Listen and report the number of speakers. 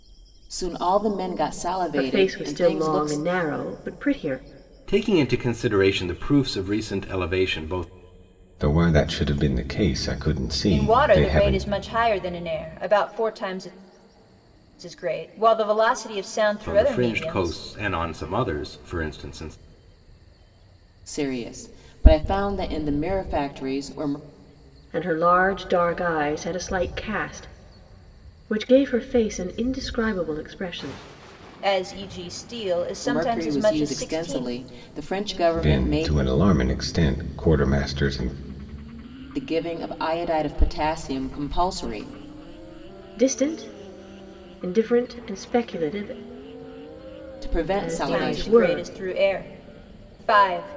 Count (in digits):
5